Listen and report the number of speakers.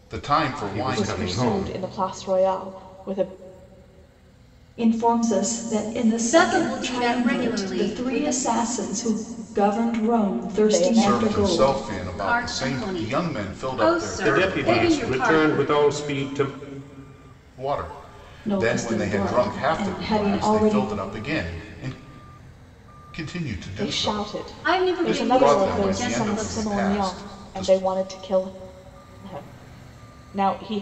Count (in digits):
5